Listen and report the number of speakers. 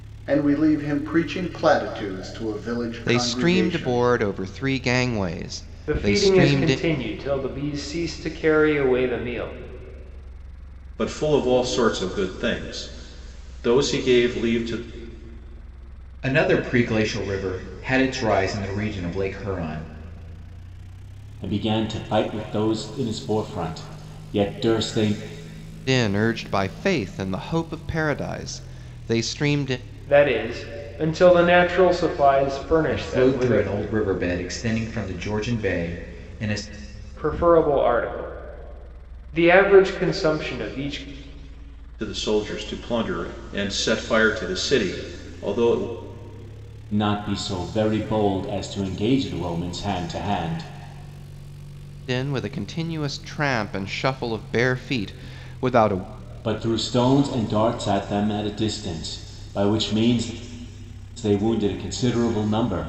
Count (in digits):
6